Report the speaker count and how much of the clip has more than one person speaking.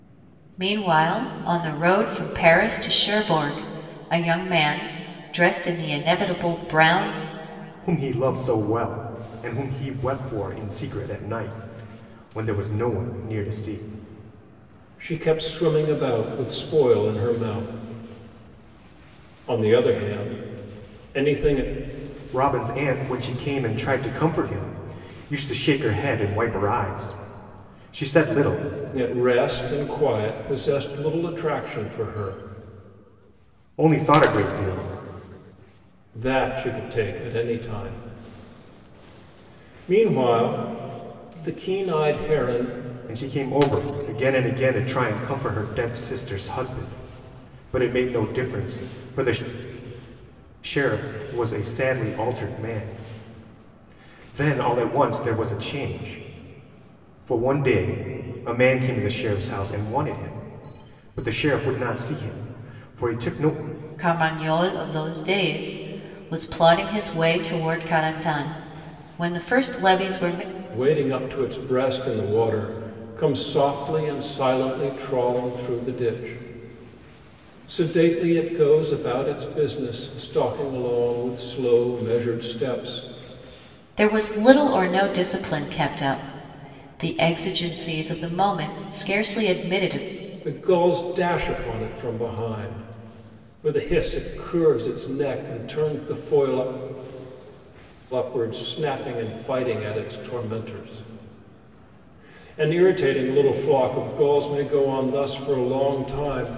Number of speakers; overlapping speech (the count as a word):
three, no overlap